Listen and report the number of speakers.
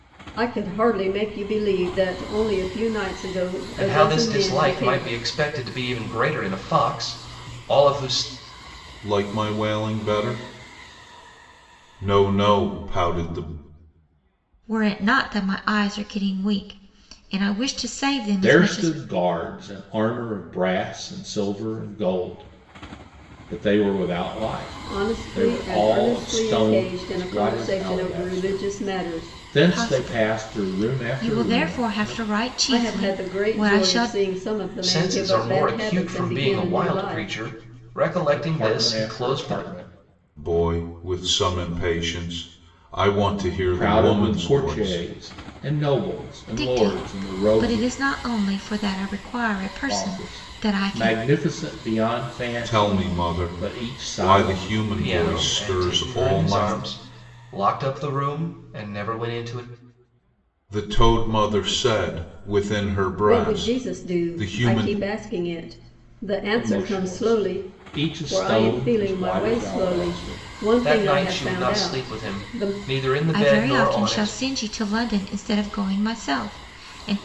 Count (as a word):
five